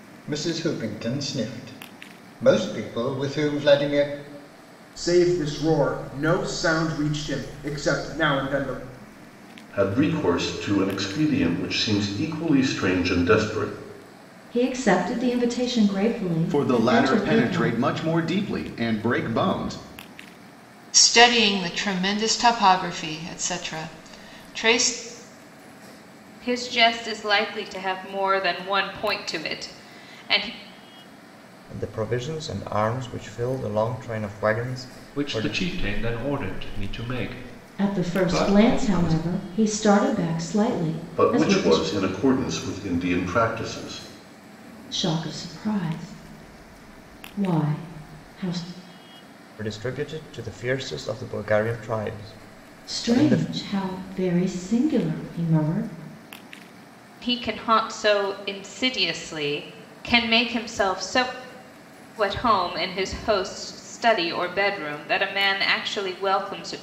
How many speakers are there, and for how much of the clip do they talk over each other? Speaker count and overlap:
nine, about 7%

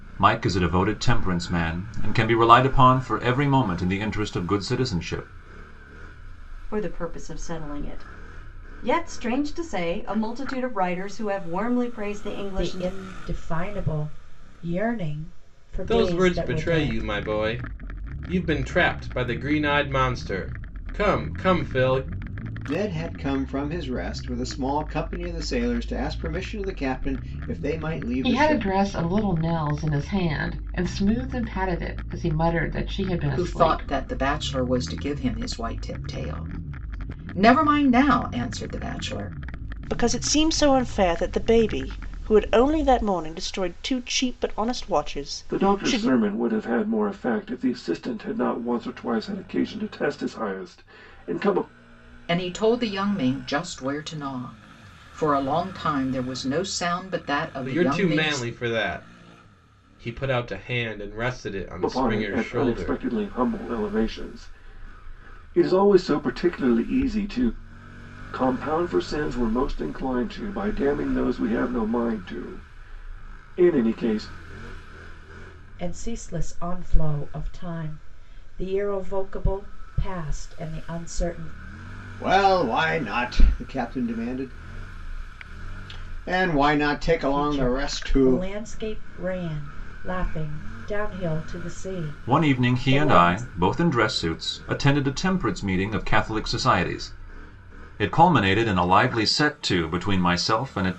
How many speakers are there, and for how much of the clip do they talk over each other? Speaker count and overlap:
nine, about 8%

